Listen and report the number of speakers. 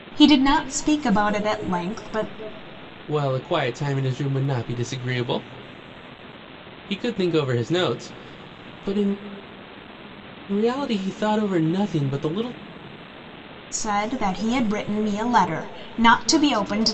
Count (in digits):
2